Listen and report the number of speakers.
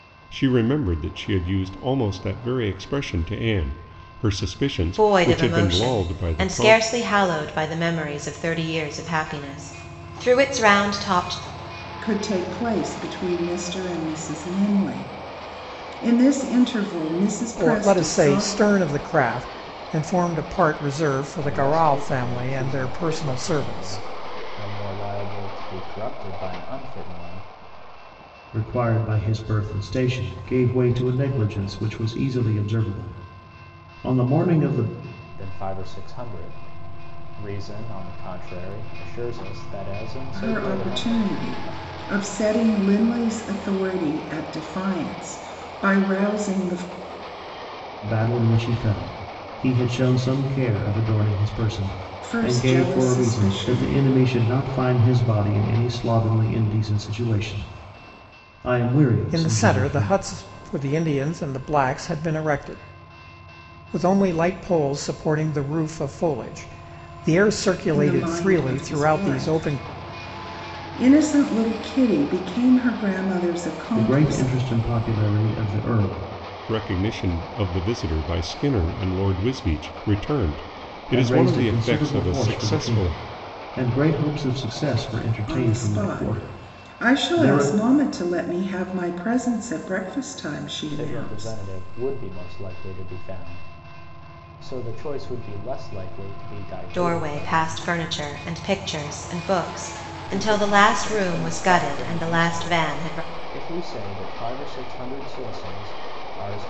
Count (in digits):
6